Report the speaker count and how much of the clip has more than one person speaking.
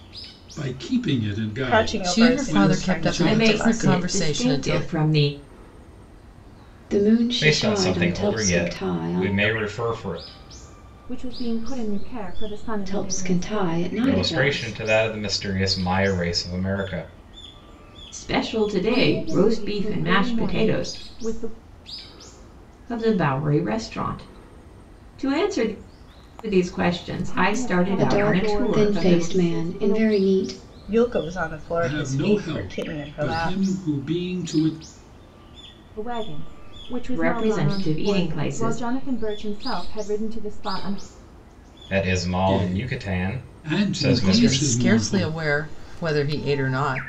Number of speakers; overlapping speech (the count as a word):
seven, about 40%